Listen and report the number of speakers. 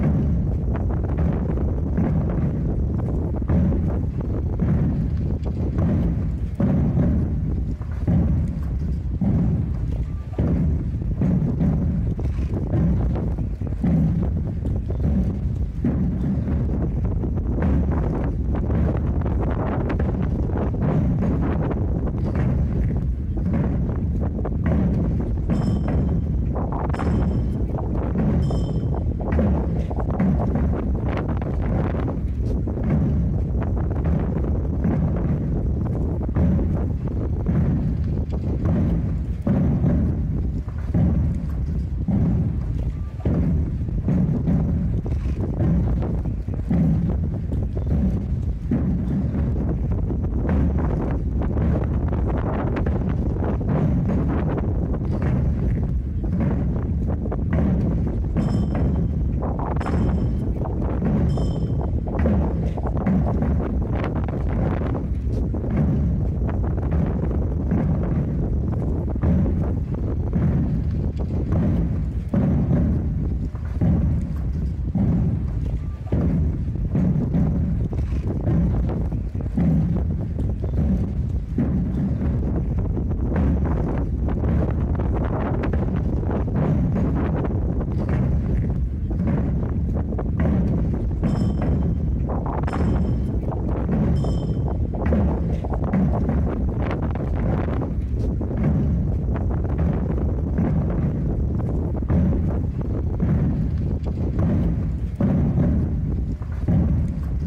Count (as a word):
zero